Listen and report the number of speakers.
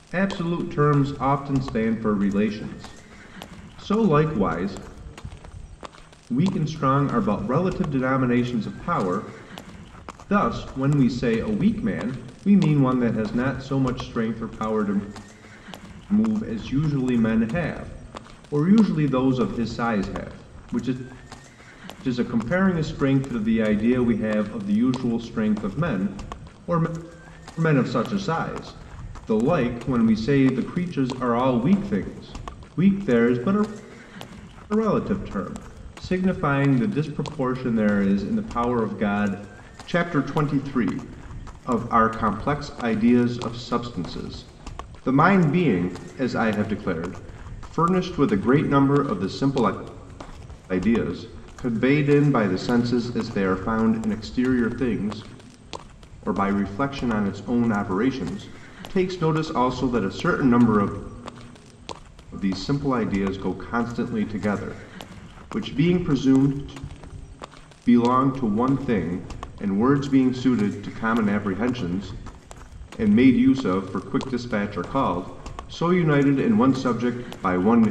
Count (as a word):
one